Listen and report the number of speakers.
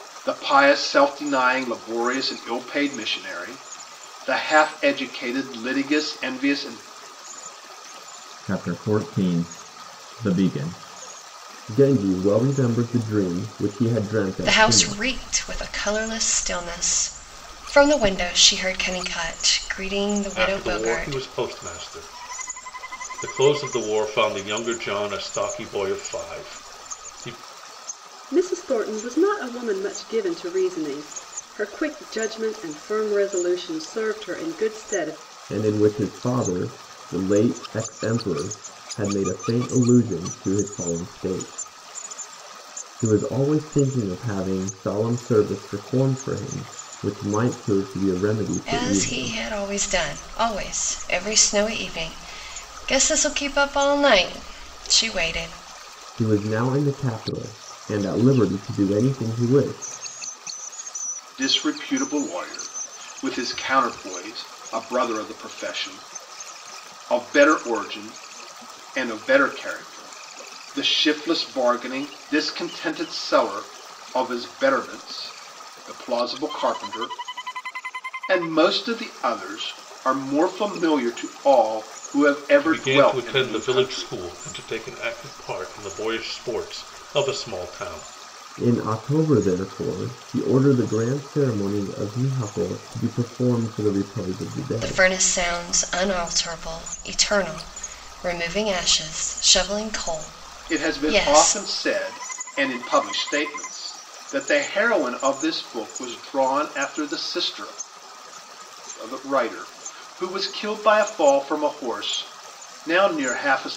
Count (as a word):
five